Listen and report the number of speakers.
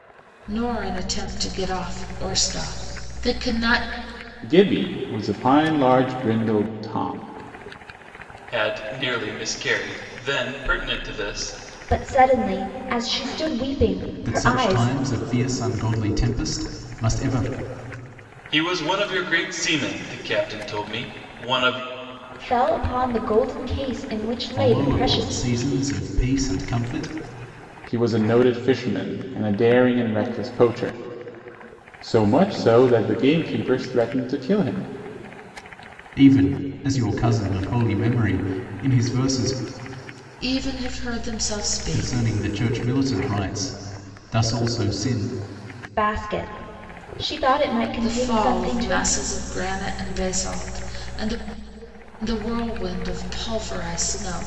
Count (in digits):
5